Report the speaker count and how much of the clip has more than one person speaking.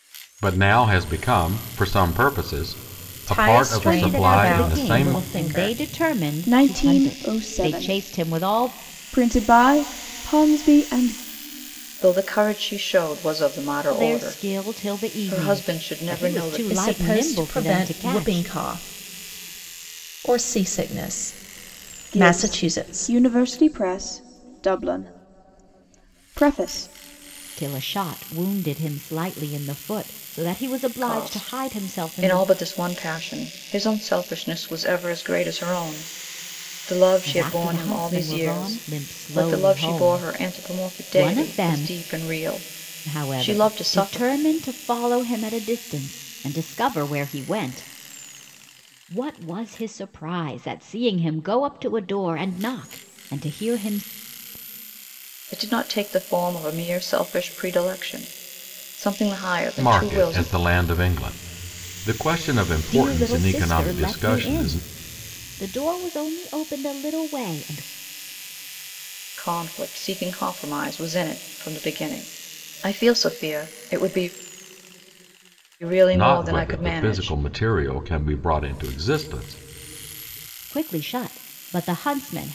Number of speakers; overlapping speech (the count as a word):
five, about 26%